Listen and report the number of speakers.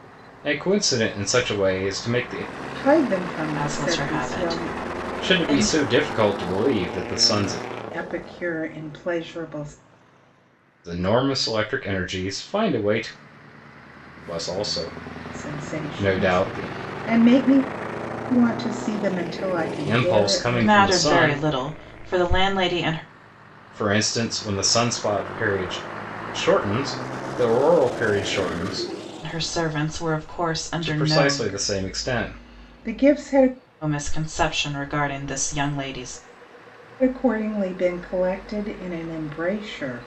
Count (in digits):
3